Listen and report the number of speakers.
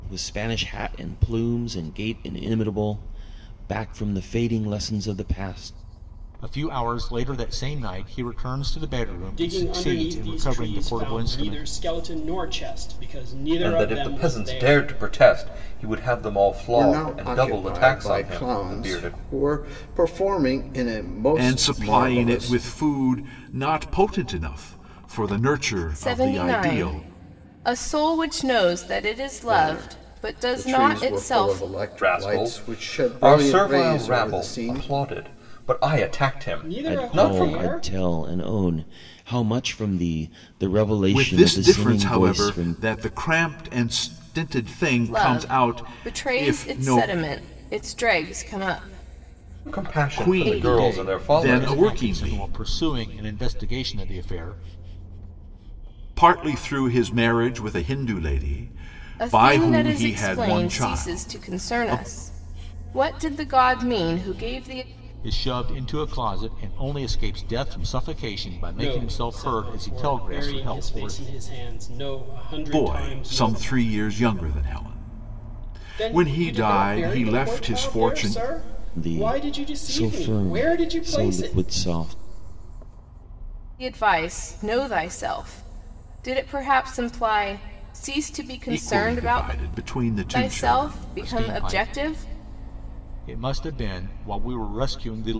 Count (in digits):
7